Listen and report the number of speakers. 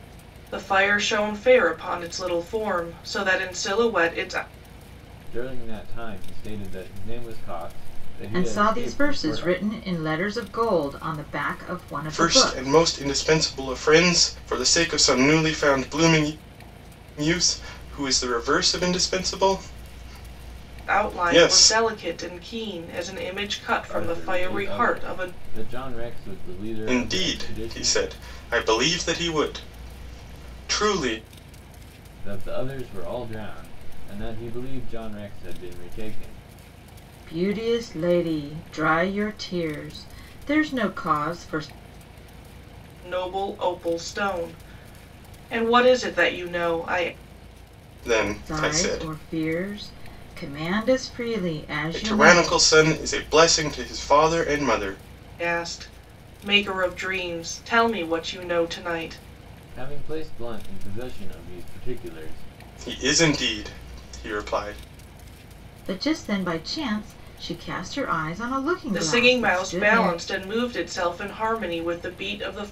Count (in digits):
4